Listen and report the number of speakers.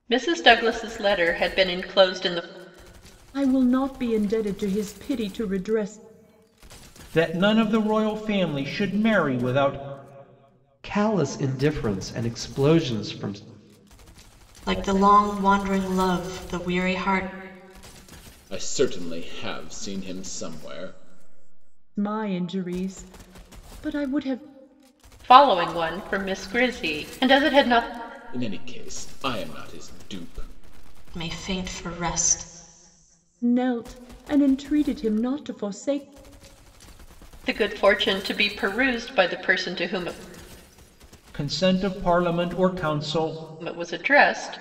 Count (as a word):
six